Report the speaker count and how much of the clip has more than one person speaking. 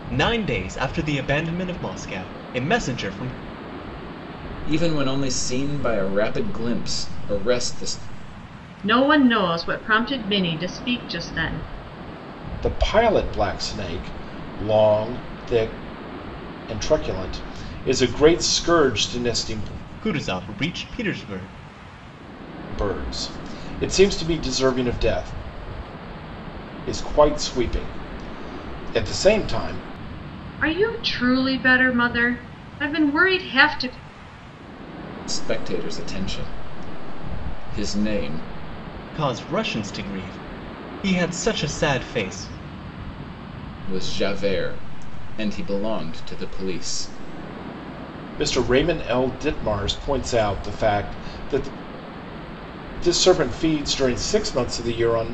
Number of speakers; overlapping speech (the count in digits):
4, no overlap